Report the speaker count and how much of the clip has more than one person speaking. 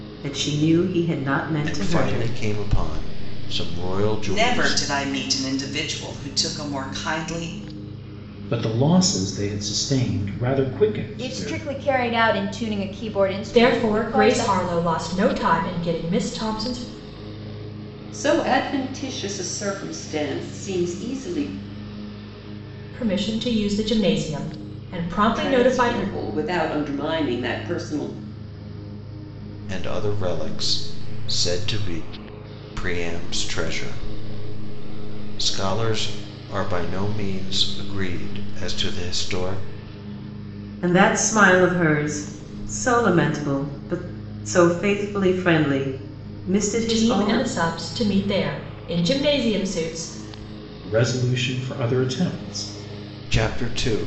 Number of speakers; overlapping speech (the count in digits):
7, about 8%